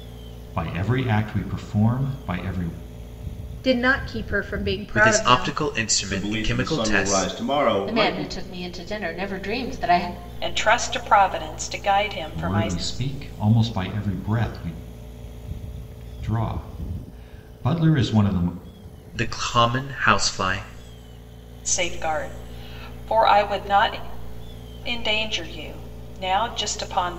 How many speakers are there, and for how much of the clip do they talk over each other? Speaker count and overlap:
six, about 11%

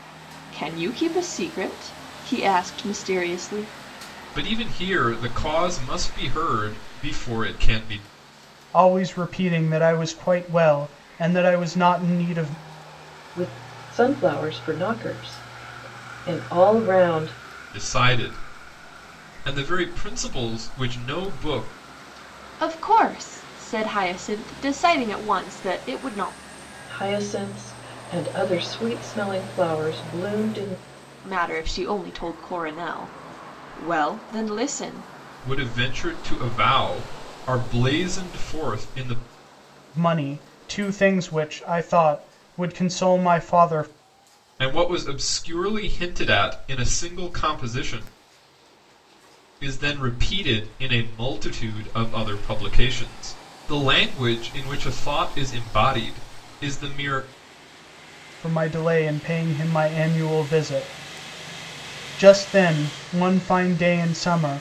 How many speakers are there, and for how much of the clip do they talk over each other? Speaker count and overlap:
four, no overlap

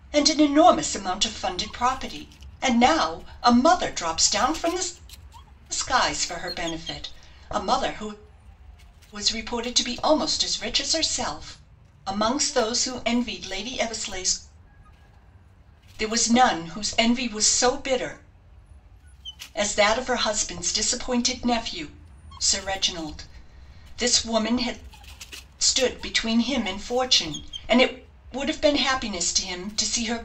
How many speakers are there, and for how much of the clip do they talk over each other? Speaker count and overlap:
one, no overlap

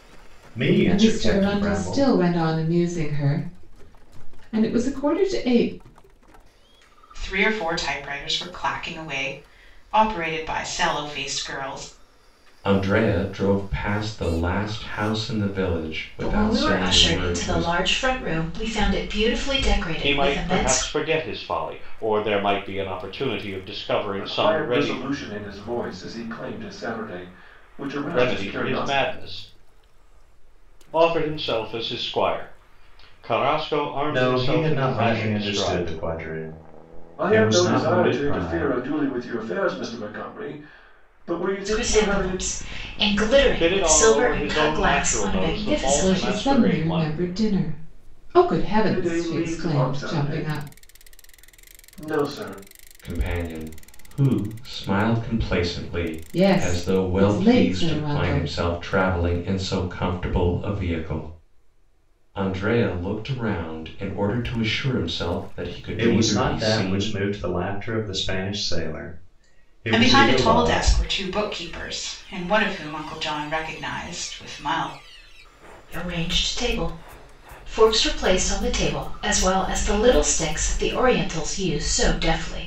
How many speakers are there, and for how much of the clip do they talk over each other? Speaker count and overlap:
seven, about 24%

